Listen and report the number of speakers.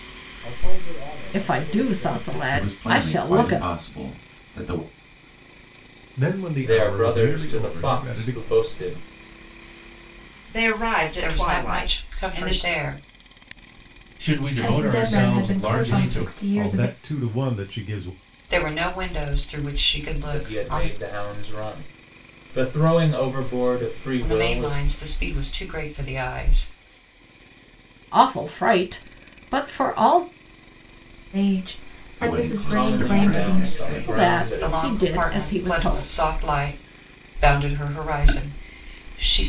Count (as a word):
nine